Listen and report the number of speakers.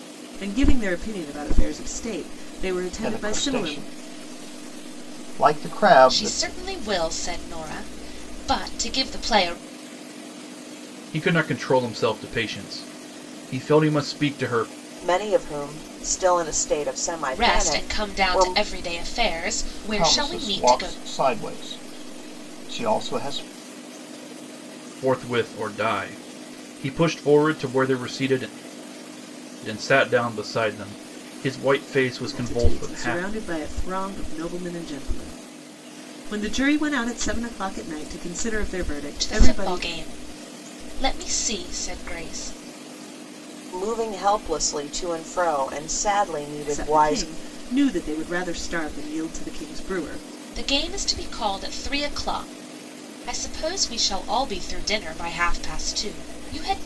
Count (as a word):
five